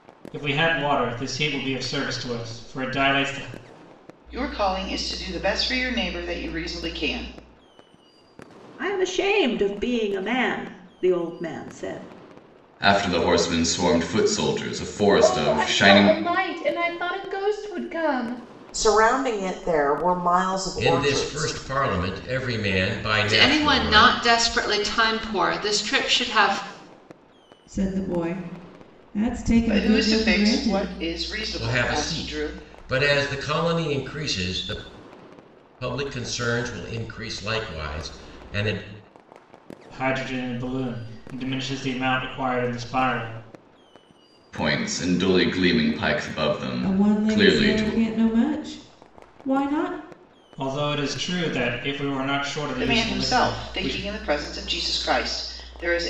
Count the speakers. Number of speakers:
9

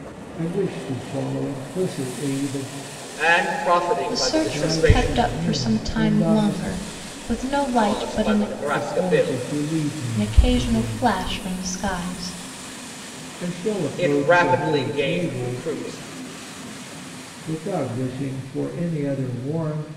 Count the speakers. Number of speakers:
3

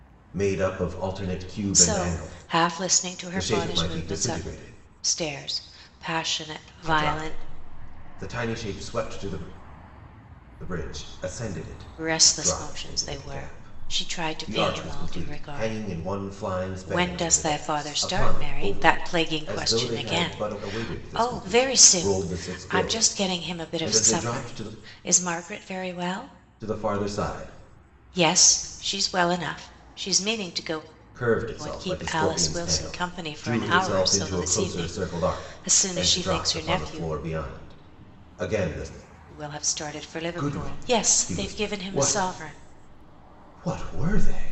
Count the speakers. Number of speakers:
2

